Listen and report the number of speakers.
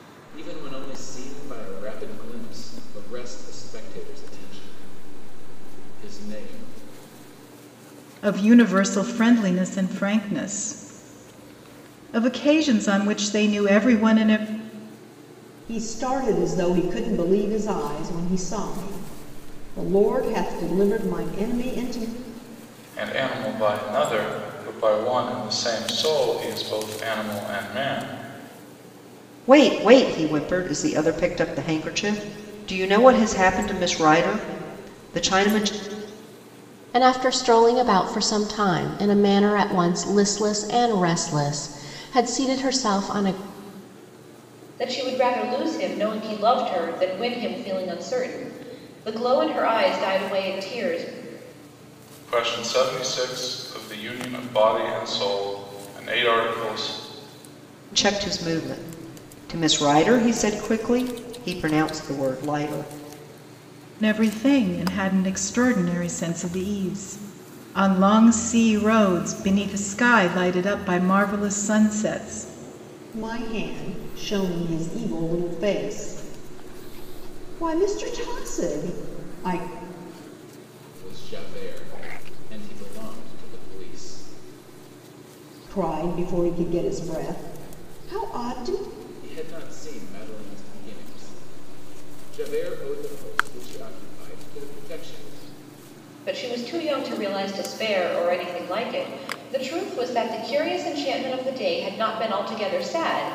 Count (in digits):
7